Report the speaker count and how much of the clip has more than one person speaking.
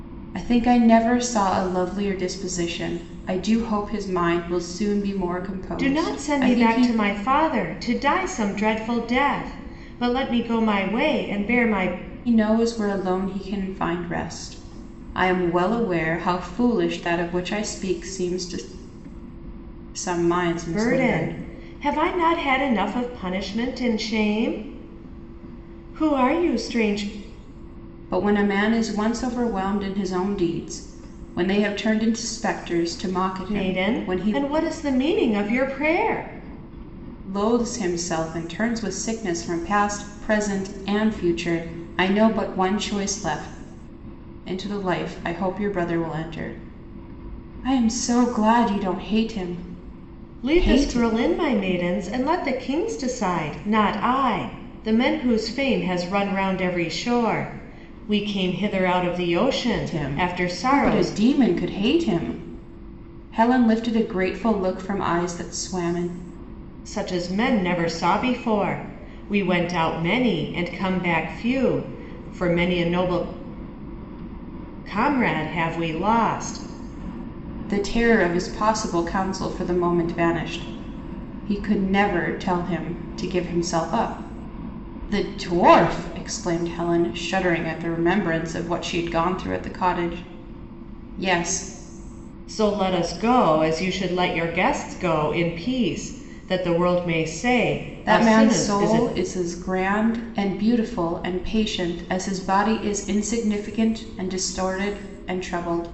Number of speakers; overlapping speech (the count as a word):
two, about 6%